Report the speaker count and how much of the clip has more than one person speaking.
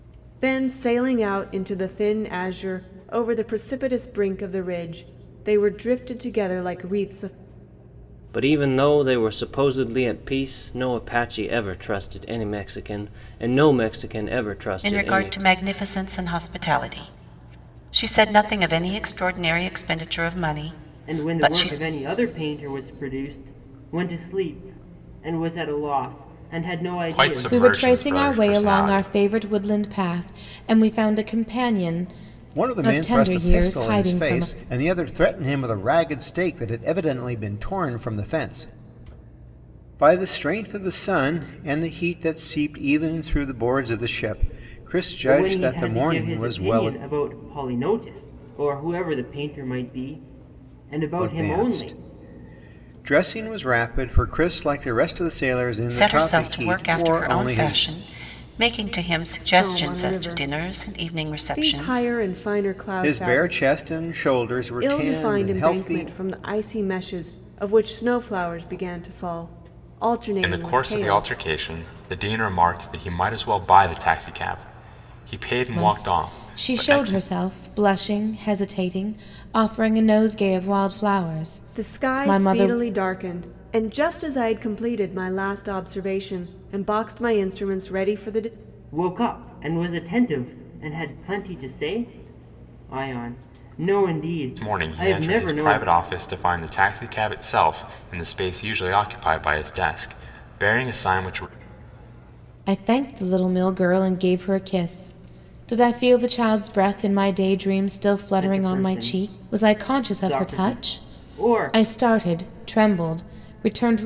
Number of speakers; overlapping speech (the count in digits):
7, about 20%